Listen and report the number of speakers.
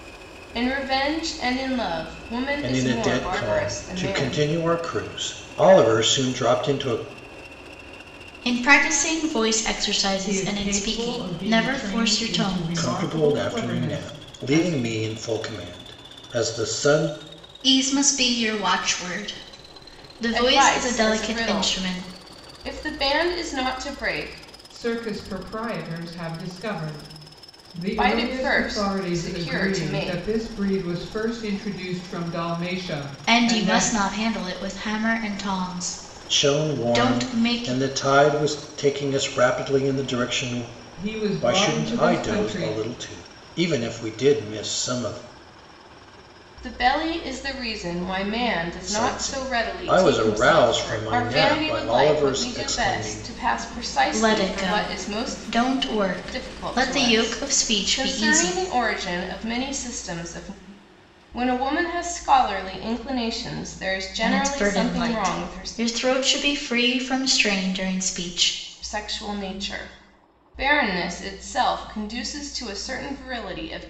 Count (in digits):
4